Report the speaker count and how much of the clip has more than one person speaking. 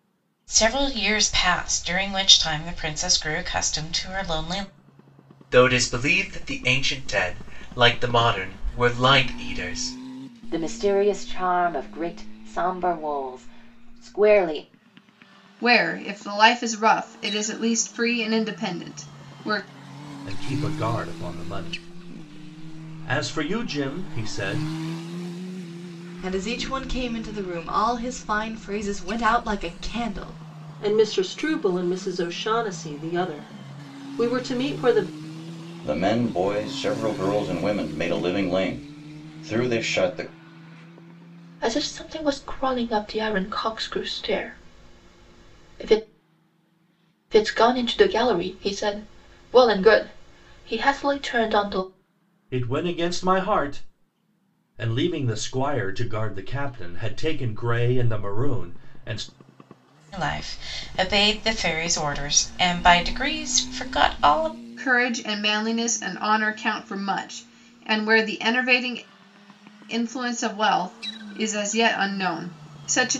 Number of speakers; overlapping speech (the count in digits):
9, no overlap